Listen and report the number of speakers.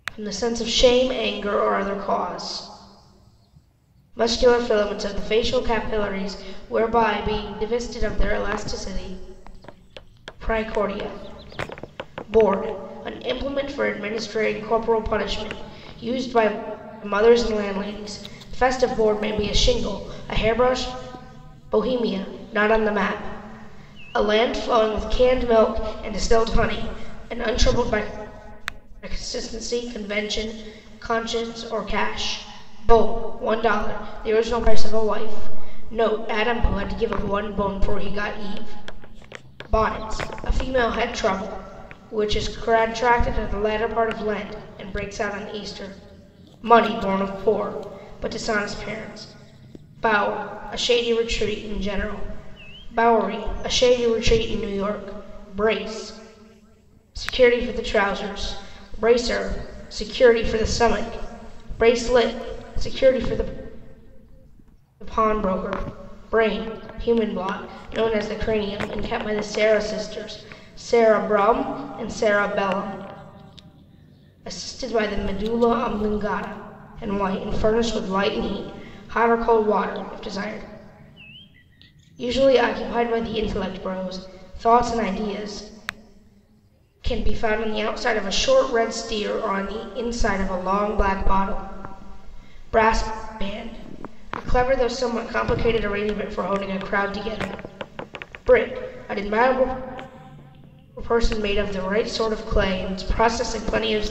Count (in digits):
1